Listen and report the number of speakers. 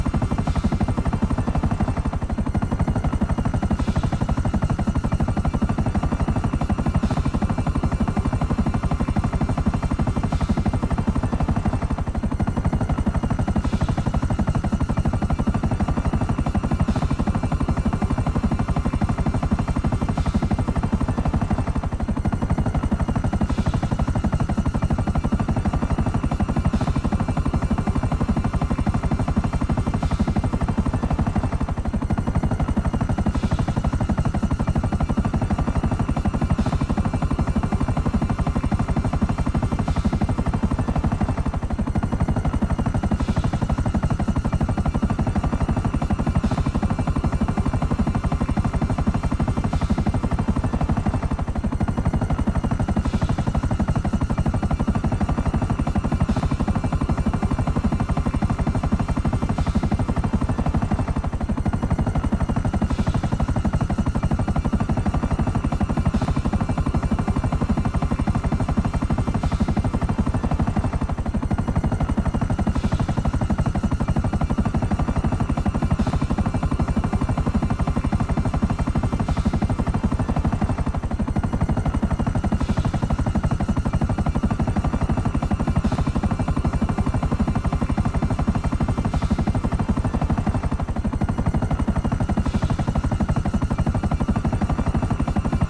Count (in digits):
0